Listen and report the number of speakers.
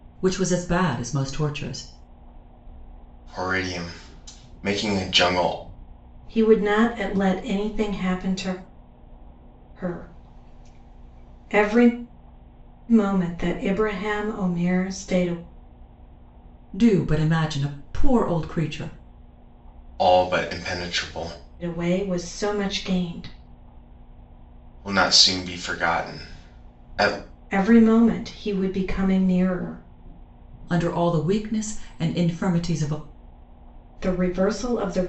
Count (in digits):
3